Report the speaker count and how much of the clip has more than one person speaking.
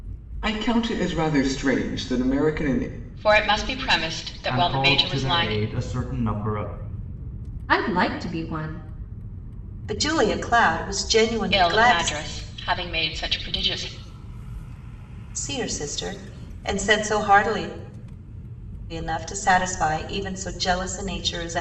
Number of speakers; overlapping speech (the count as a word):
five, about 8%